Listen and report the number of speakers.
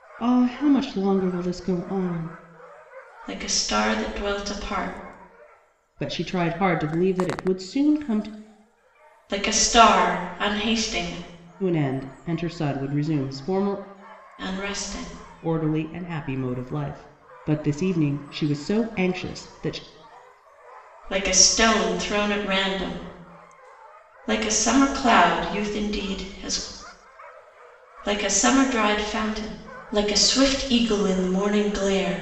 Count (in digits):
2